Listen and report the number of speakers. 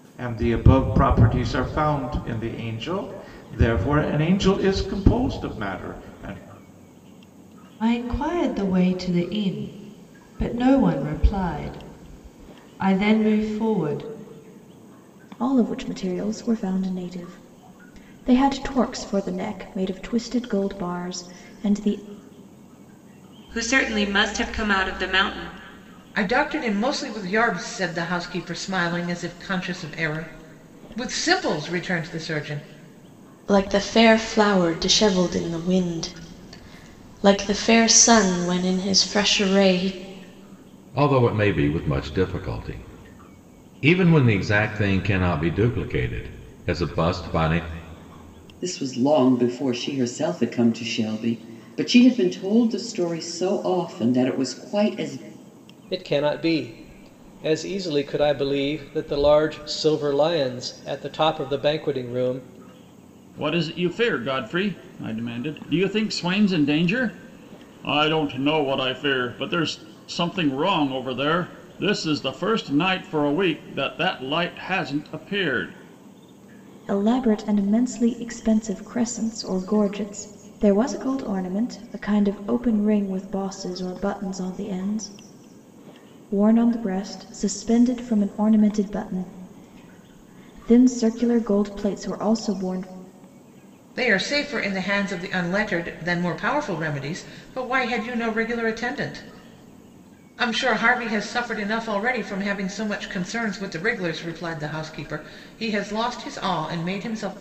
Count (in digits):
10